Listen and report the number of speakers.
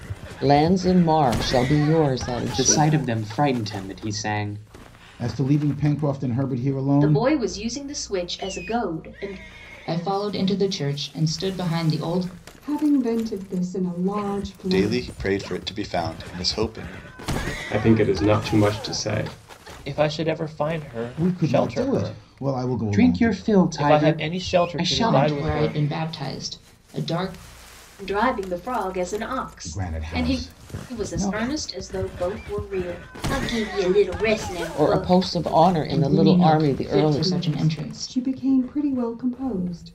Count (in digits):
9